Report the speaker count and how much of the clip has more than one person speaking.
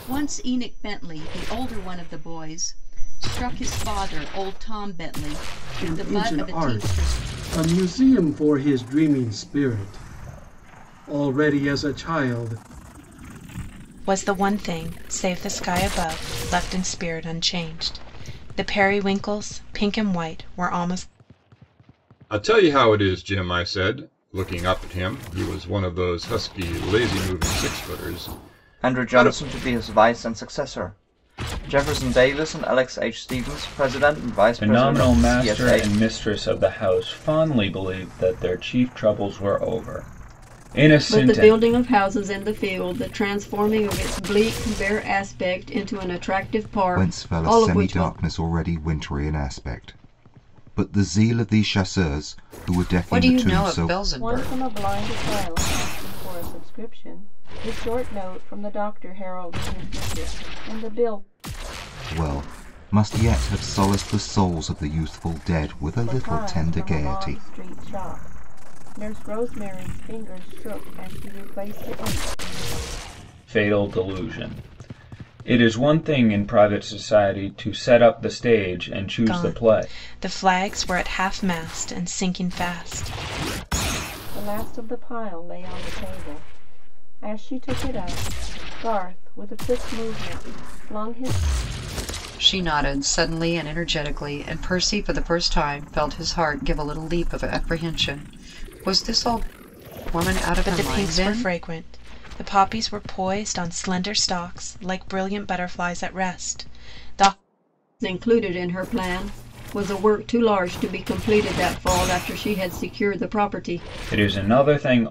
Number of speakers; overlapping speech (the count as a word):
ten, about 8%